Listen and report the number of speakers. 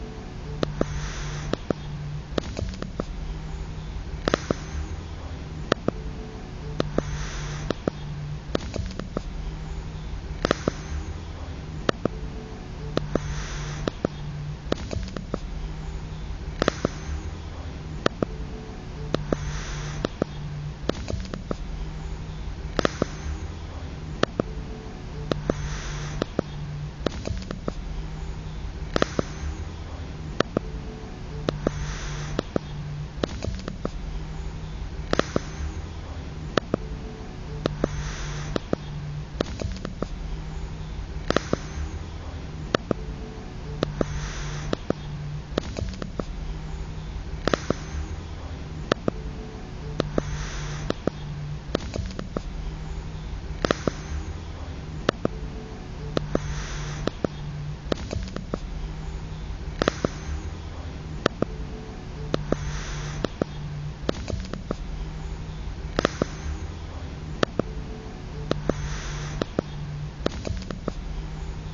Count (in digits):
0